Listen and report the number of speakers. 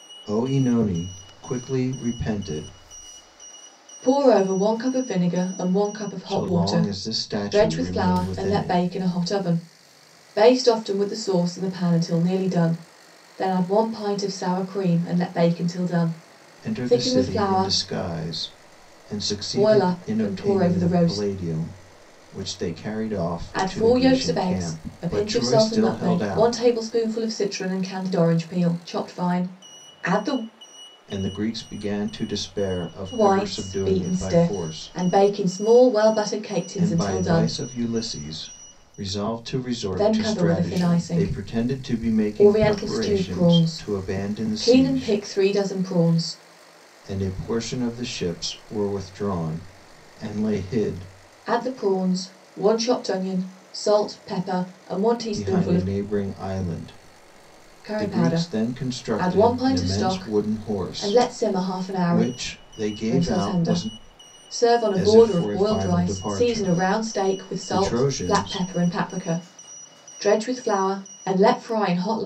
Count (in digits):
2